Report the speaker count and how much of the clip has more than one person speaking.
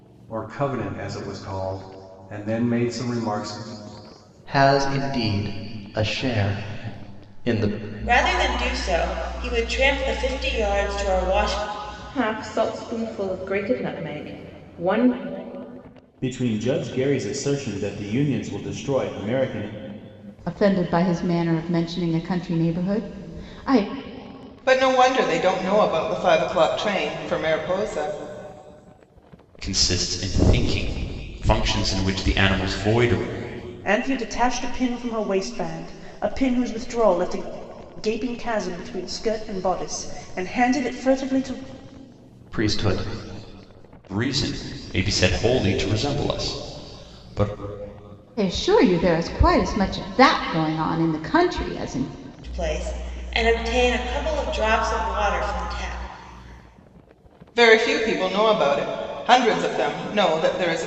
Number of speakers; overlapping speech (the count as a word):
nine, no overlap